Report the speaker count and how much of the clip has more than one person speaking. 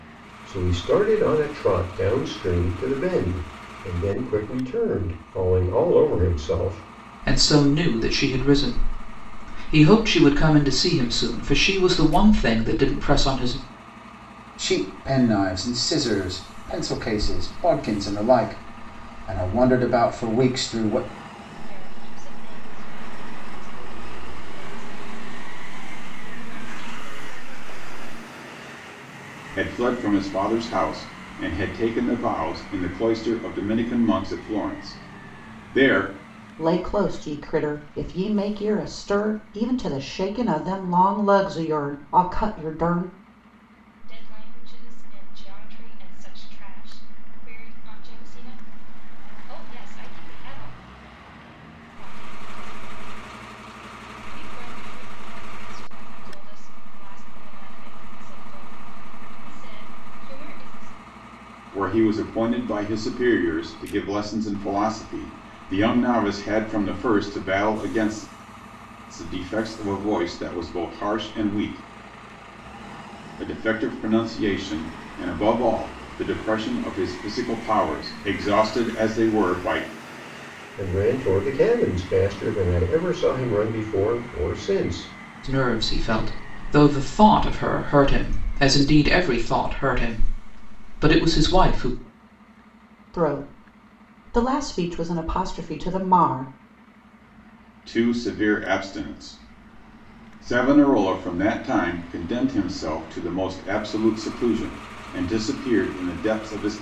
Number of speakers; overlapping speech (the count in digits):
6, no overlap